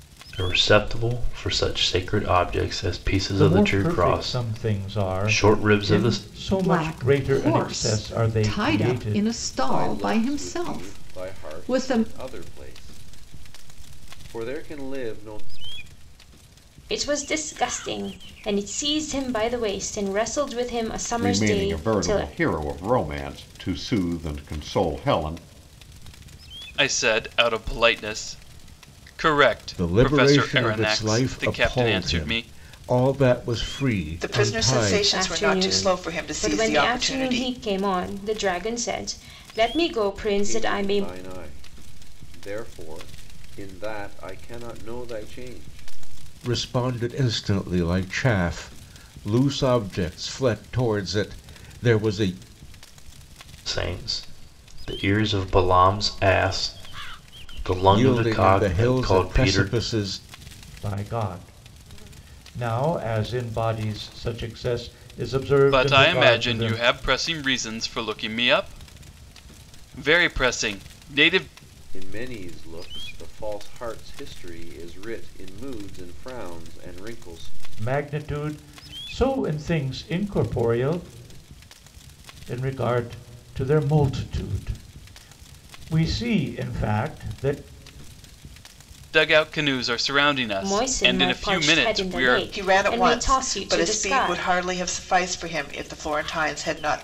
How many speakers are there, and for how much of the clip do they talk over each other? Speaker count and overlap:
9, about 24%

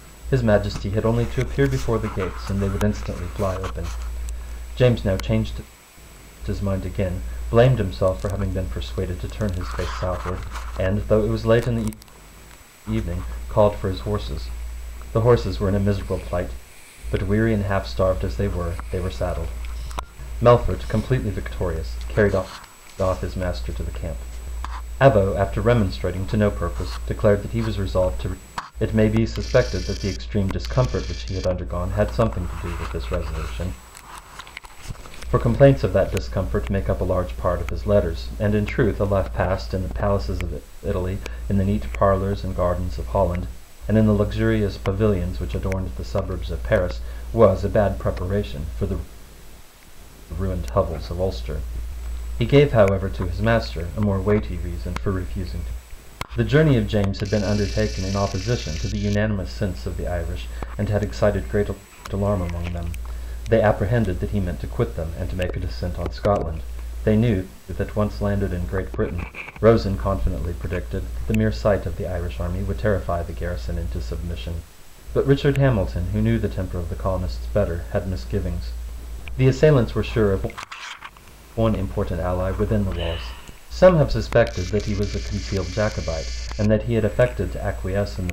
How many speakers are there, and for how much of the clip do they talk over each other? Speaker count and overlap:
1, no overlap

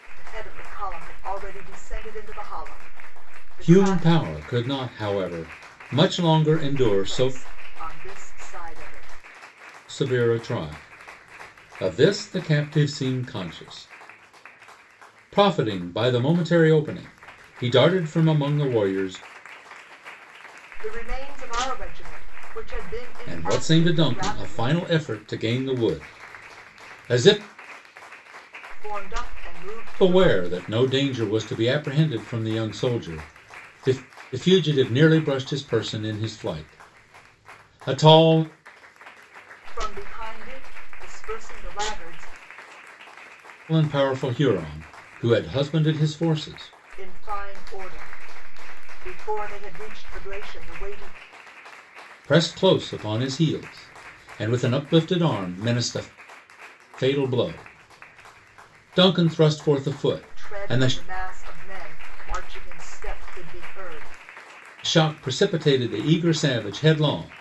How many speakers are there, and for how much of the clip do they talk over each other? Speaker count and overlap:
2, about 6%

